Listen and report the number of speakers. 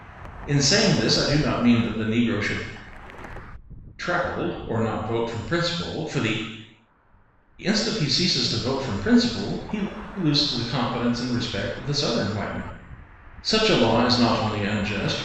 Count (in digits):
1